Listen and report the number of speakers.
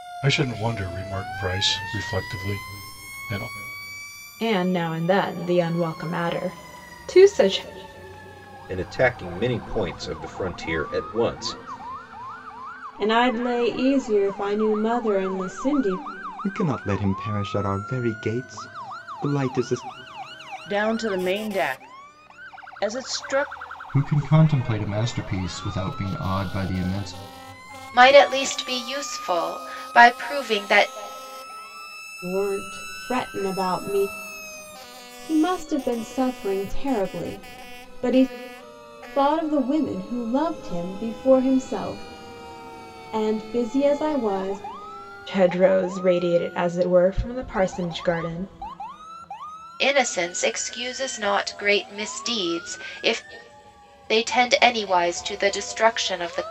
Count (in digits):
8